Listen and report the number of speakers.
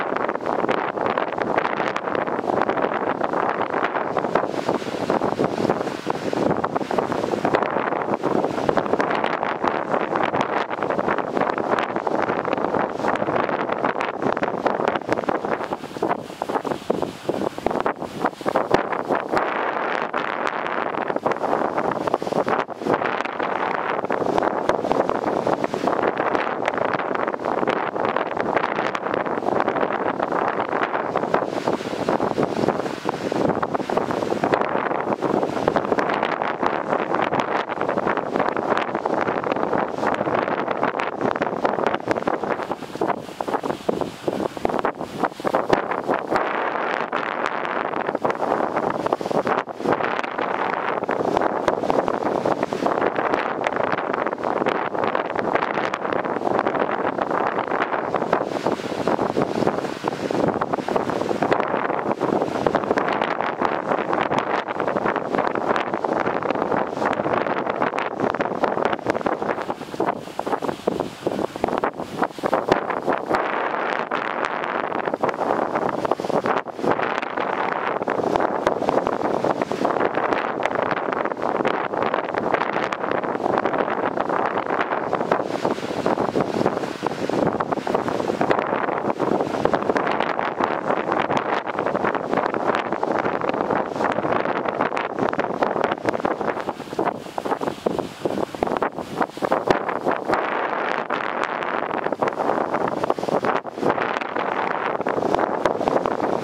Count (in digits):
0